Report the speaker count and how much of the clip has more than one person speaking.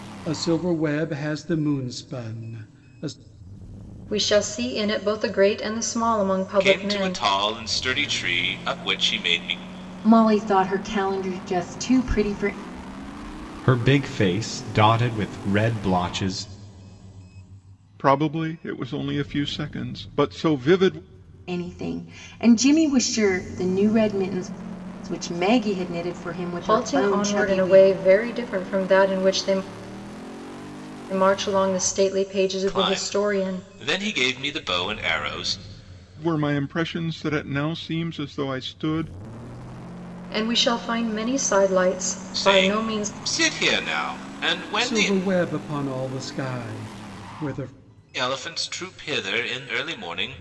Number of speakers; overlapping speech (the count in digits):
6, about 8%